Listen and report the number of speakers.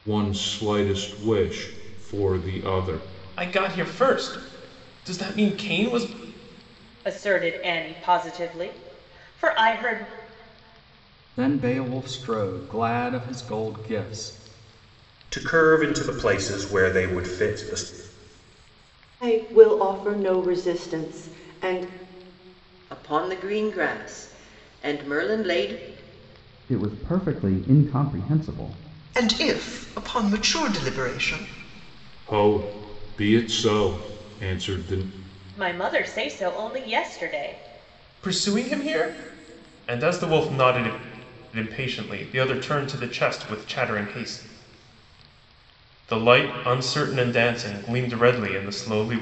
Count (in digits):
9